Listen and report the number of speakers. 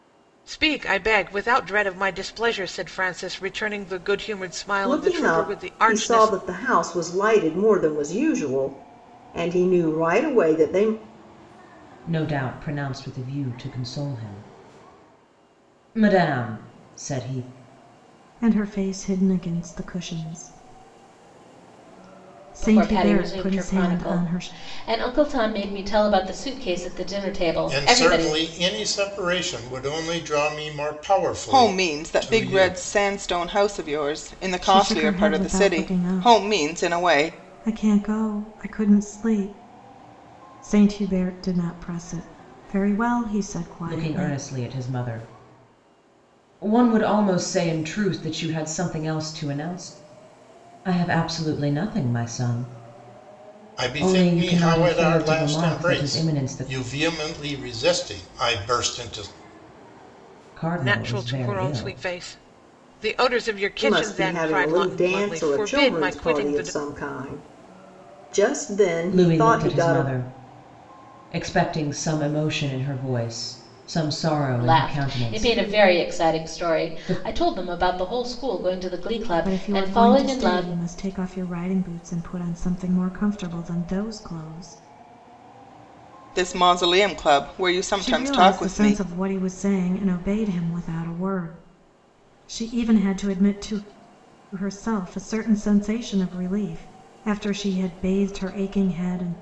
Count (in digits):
7